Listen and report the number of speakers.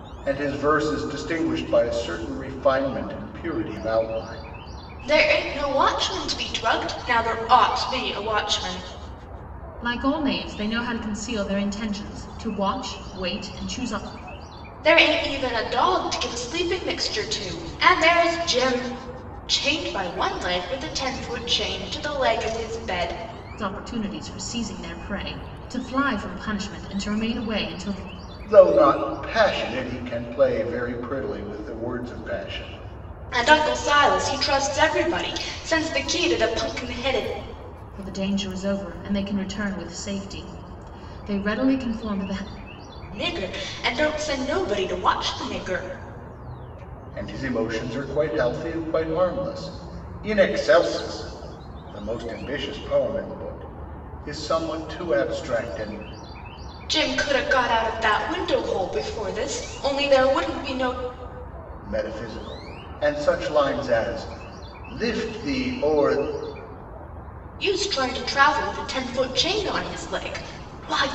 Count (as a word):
three